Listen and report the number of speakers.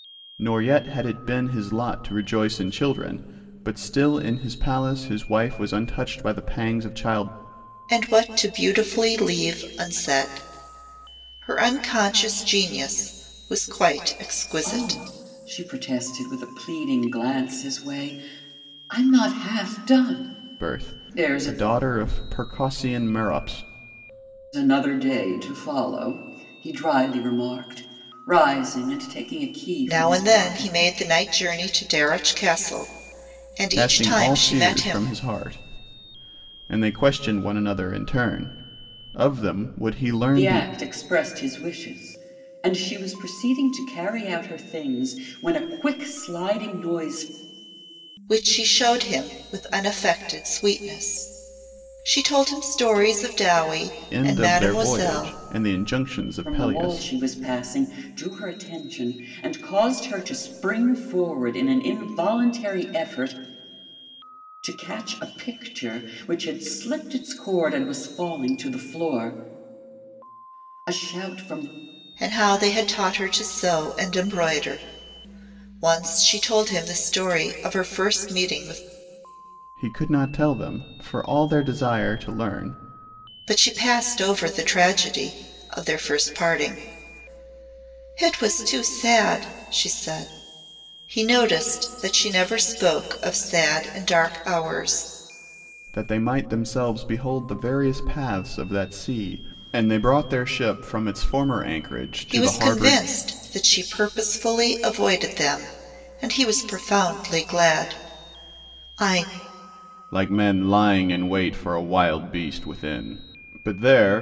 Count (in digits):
3